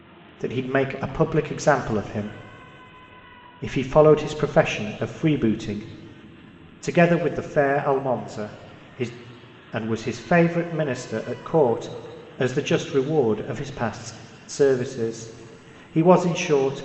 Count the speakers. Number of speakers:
1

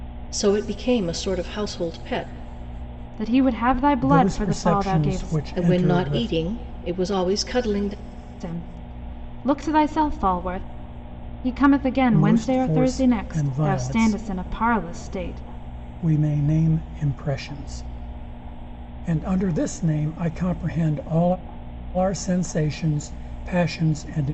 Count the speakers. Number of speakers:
3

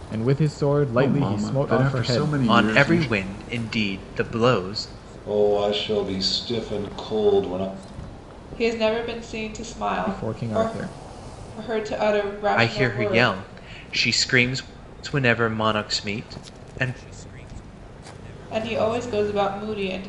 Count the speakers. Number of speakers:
5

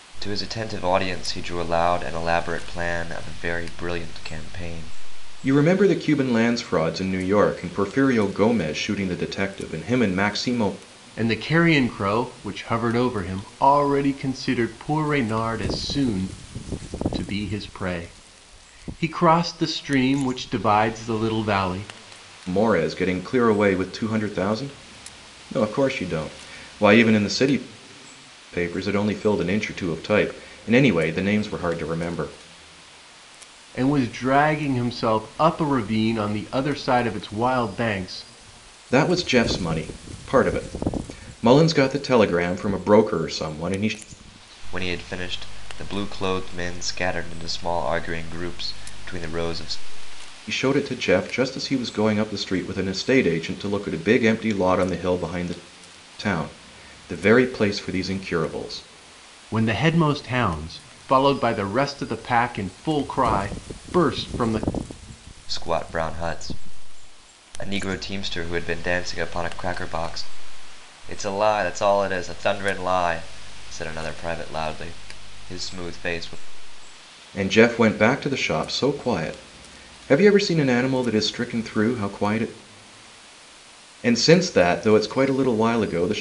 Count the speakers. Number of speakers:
3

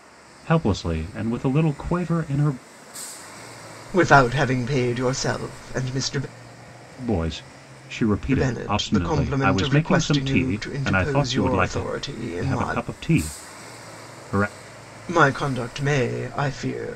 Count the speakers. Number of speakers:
2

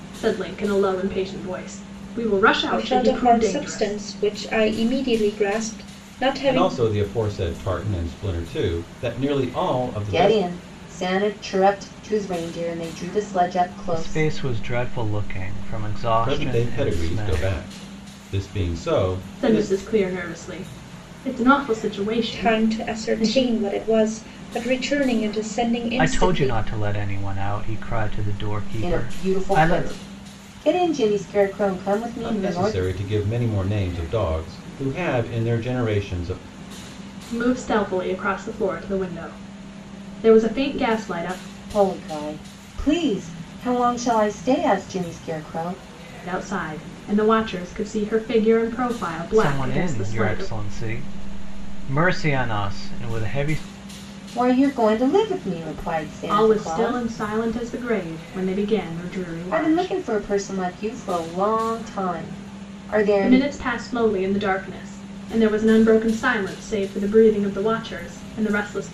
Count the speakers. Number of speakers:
5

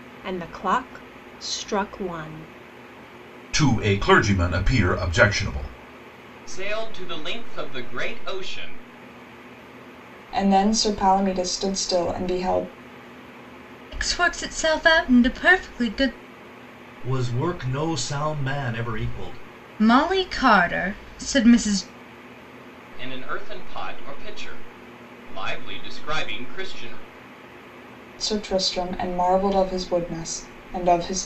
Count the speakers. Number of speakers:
6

